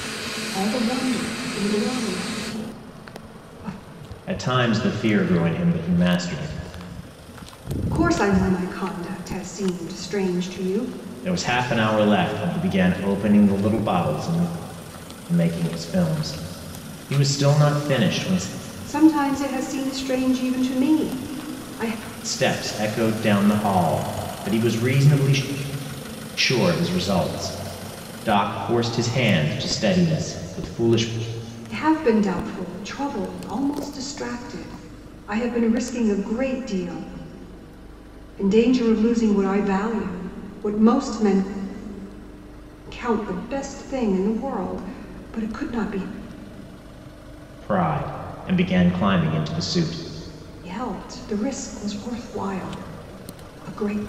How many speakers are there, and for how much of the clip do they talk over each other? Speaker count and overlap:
2, no overlap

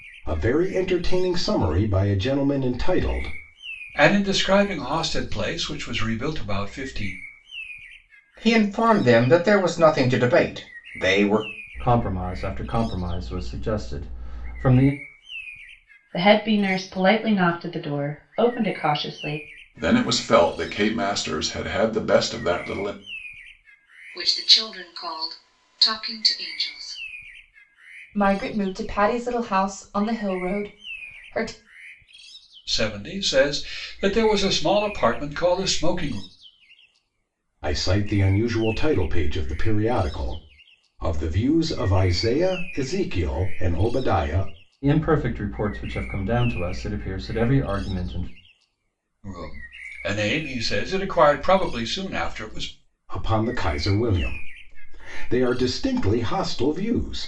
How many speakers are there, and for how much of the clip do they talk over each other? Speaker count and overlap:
8, no overlap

